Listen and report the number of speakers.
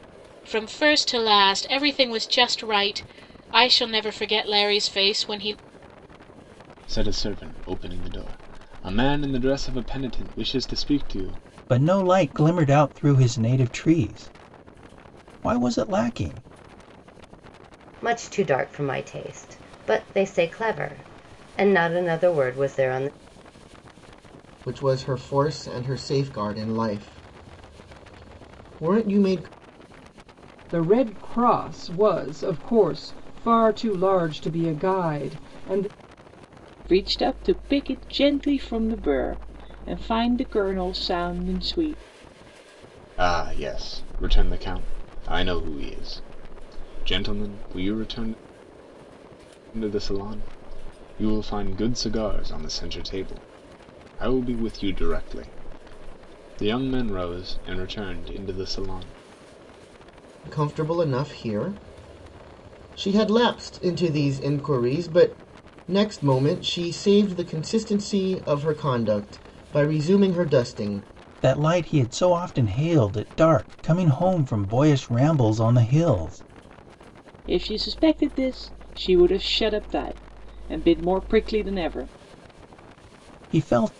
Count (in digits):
7